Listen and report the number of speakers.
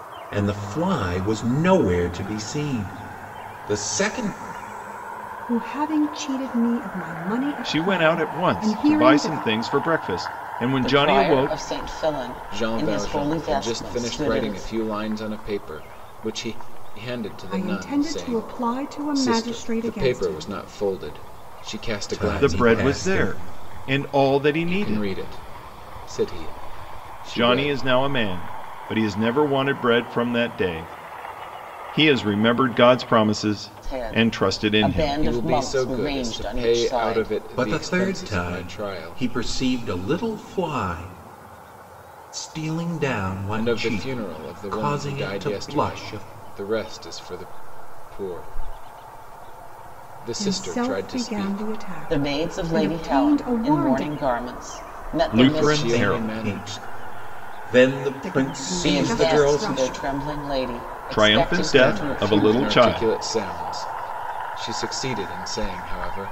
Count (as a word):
five